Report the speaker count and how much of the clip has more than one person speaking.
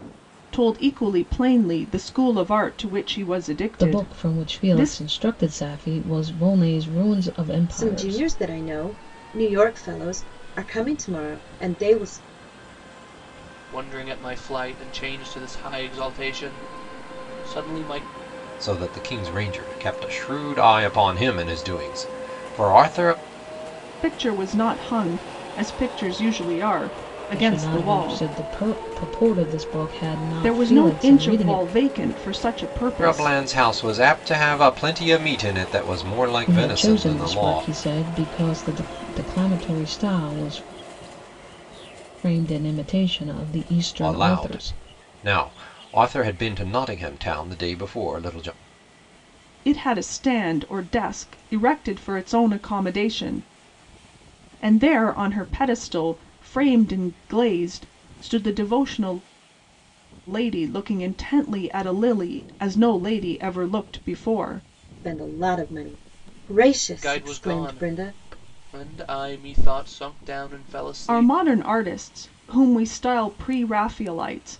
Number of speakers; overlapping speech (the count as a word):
five, about 11%